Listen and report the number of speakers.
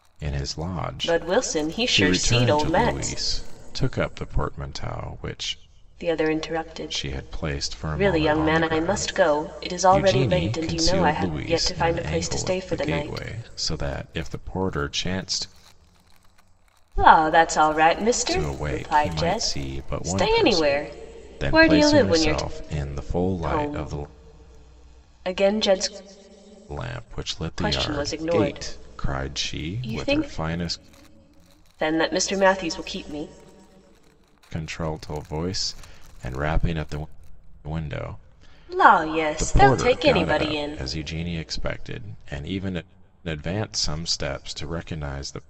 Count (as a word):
two